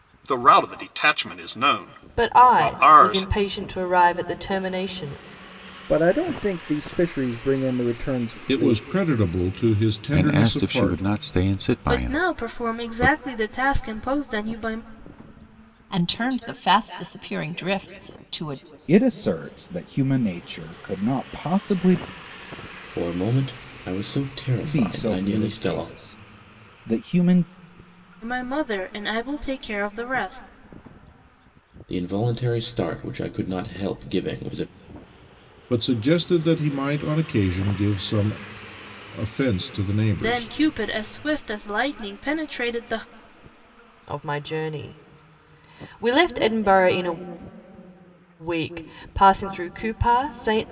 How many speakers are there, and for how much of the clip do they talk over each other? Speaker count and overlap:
9, about 11%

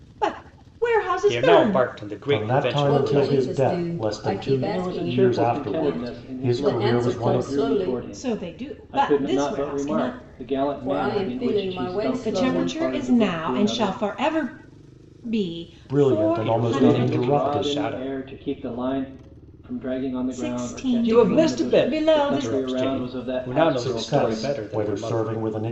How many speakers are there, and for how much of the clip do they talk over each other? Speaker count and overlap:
5, about 75%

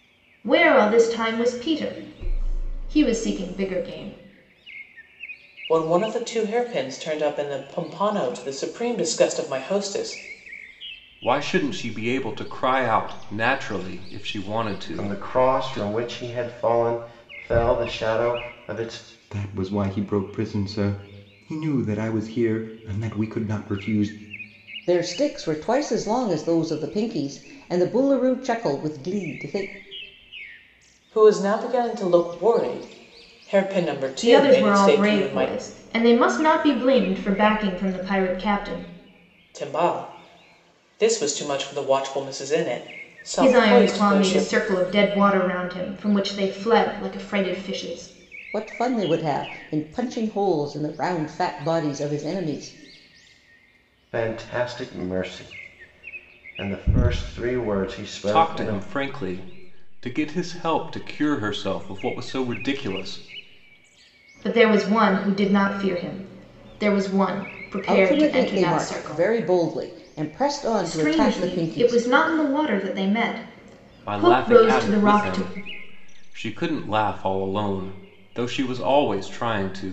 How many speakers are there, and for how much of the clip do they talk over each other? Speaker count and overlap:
6, about 10%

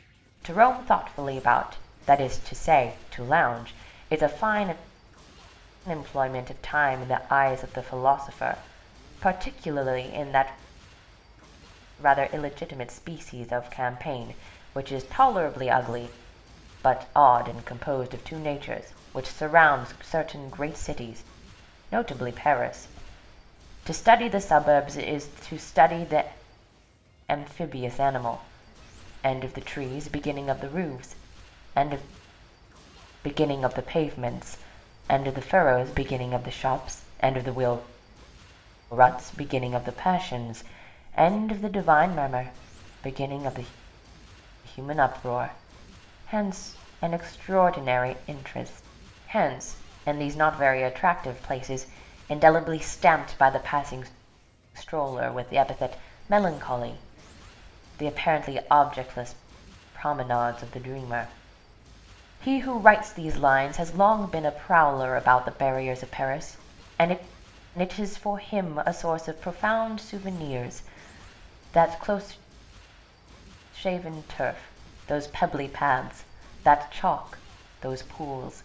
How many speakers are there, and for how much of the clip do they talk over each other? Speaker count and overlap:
1, no overlap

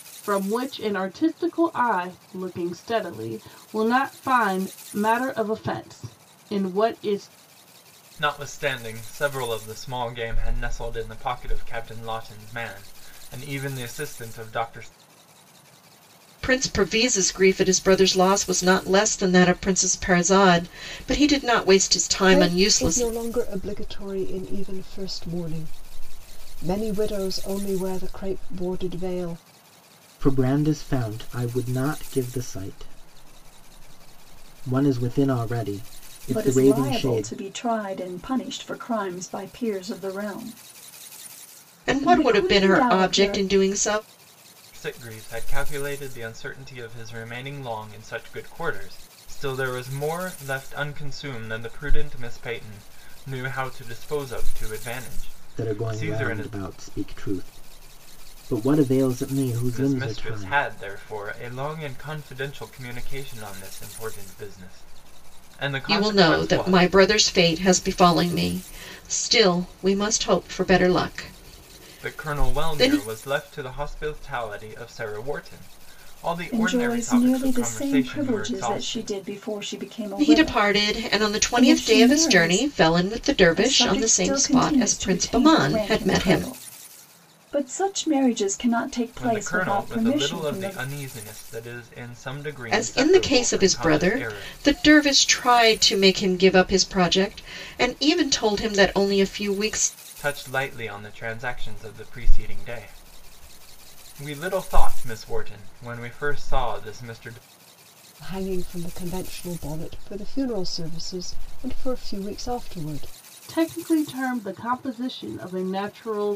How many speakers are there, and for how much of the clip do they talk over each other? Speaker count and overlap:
6, about 17%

